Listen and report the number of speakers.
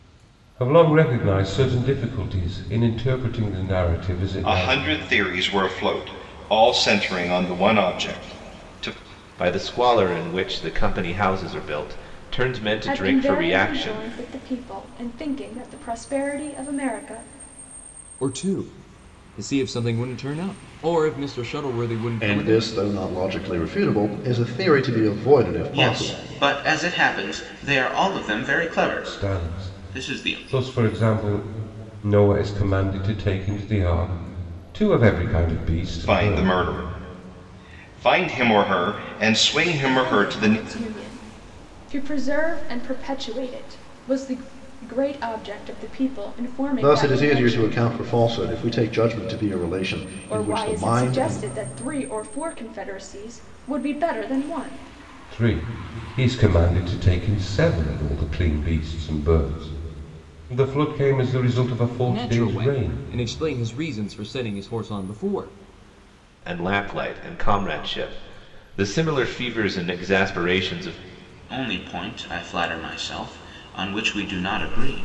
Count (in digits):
7